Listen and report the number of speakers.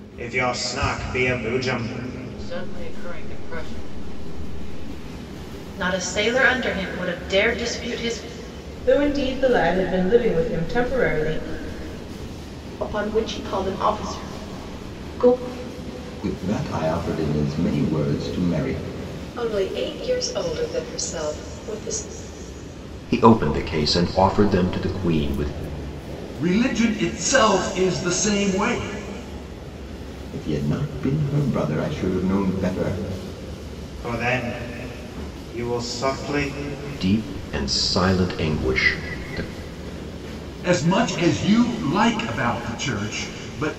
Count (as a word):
nine